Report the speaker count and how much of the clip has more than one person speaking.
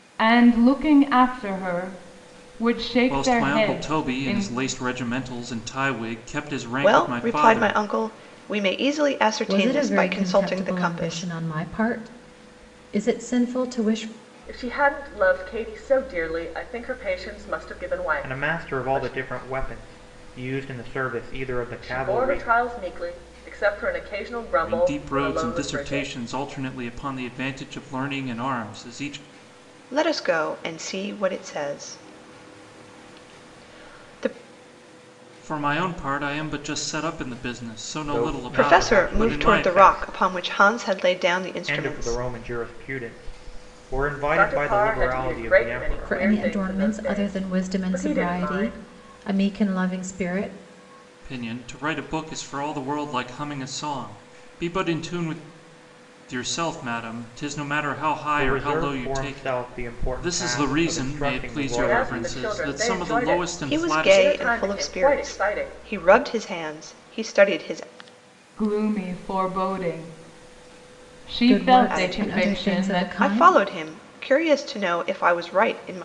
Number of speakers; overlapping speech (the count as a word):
six, about 32%